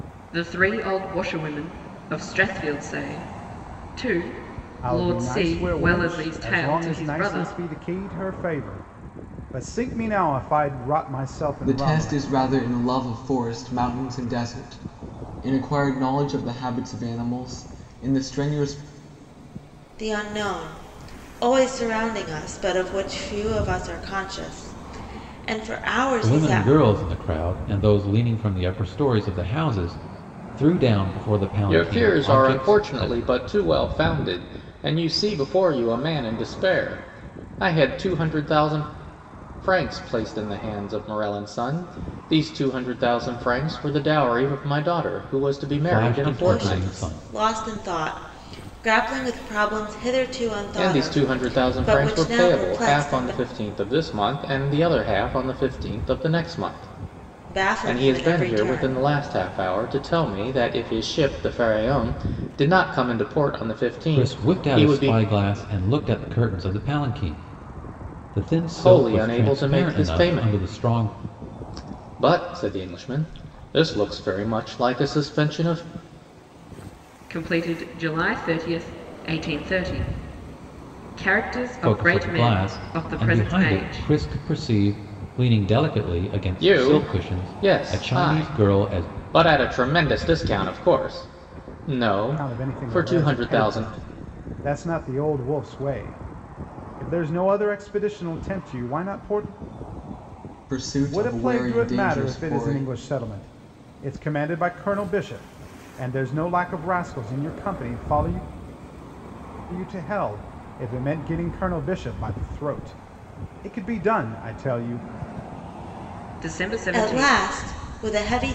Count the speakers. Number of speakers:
6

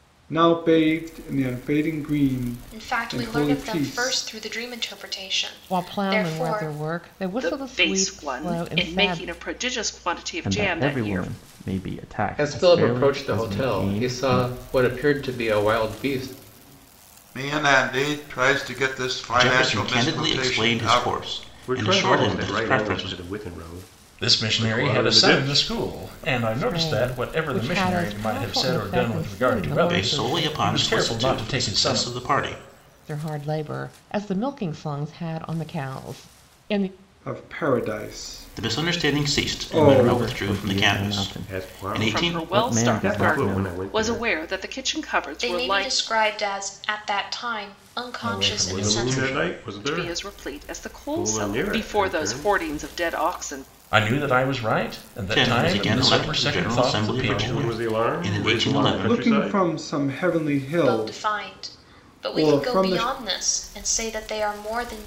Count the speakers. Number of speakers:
10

